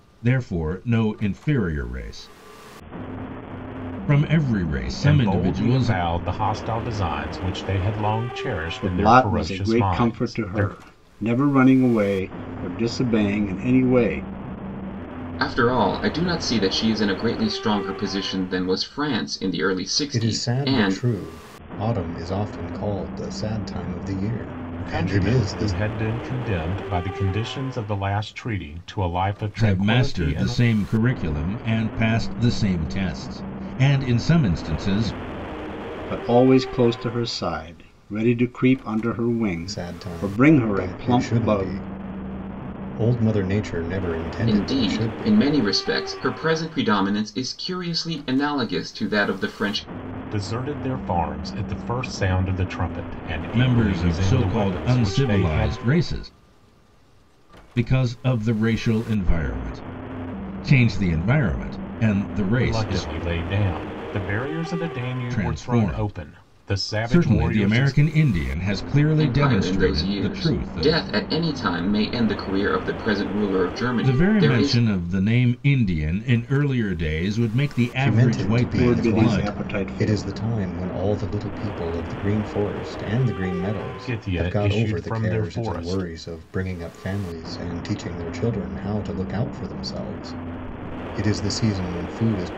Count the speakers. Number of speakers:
five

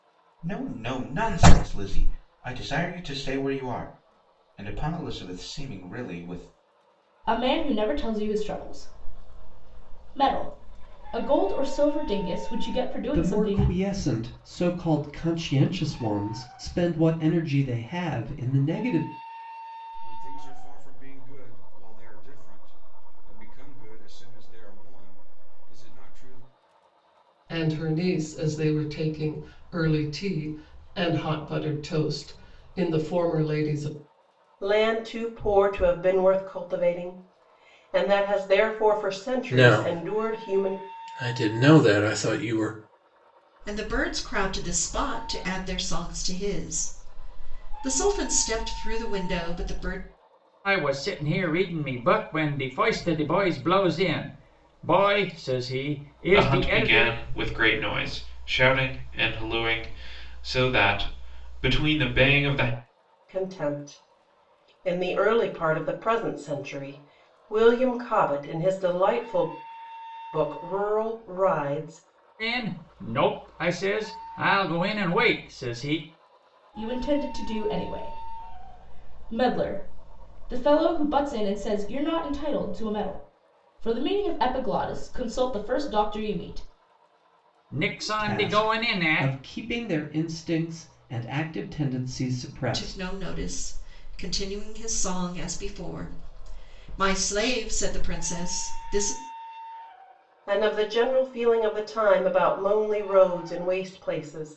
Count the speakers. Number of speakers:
ten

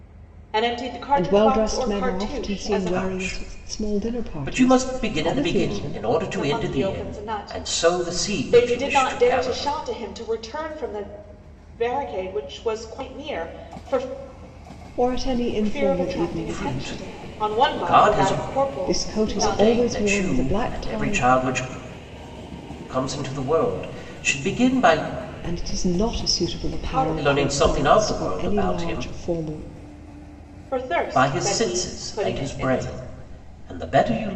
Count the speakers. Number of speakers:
three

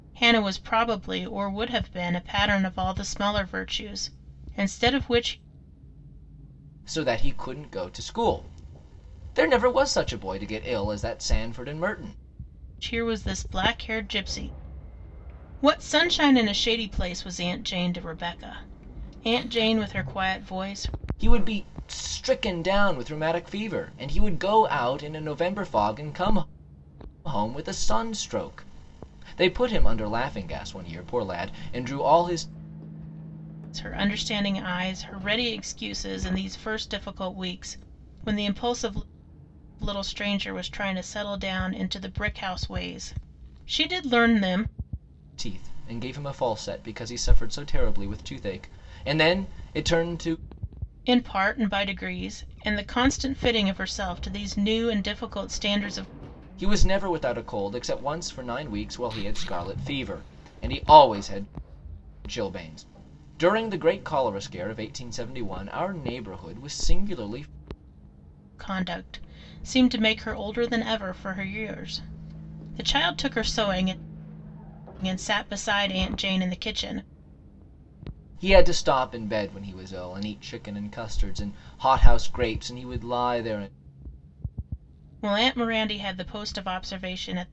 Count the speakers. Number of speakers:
two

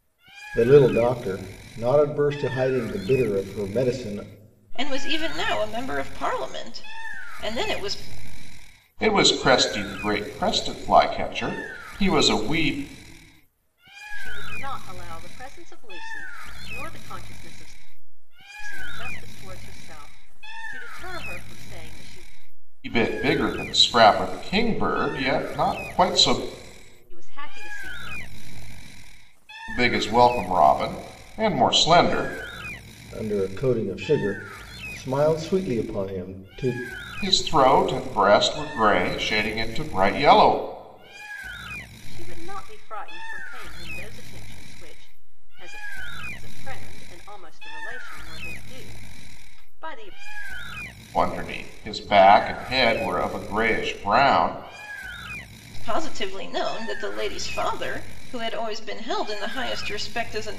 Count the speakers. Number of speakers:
four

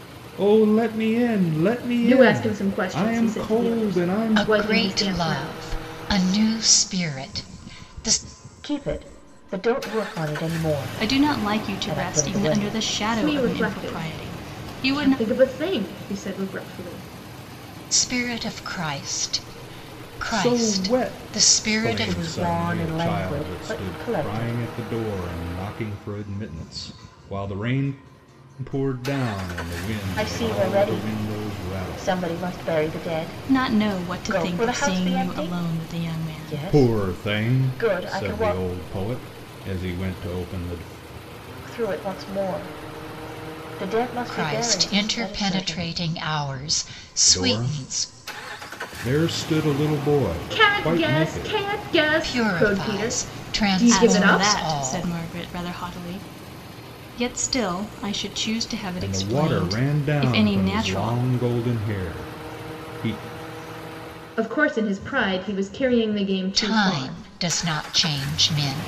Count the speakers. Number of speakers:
five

